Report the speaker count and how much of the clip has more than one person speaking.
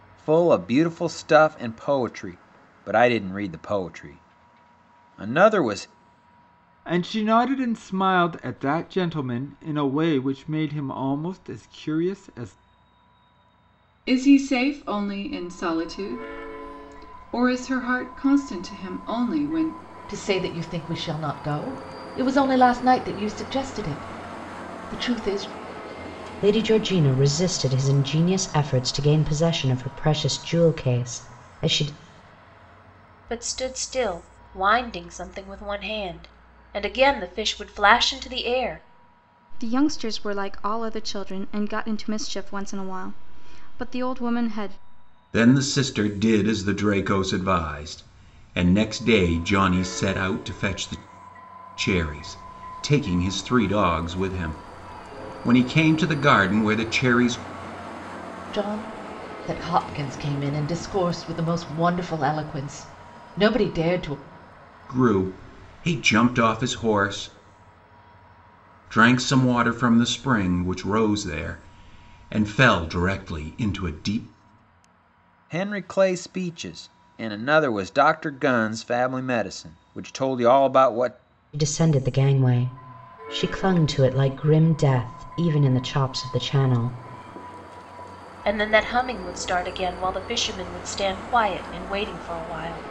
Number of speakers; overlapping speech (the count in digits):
8, no overlap